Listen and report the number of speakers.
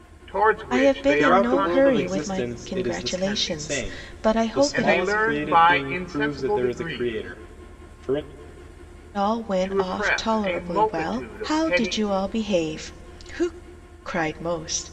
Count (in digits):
3